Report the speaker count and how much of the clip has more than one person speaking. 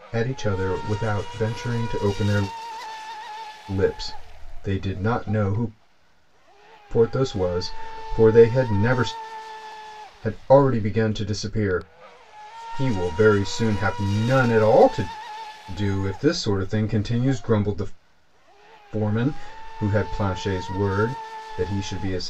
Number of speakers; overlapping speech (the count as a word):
one, no overlap